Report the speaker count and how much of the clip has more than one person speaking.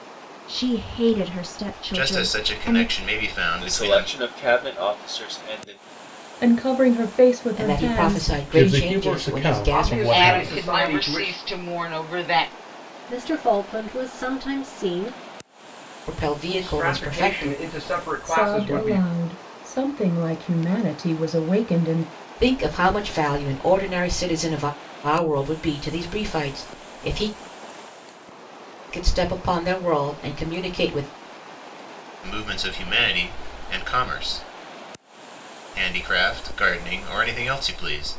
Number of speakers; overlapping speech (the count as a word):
nine, about 19%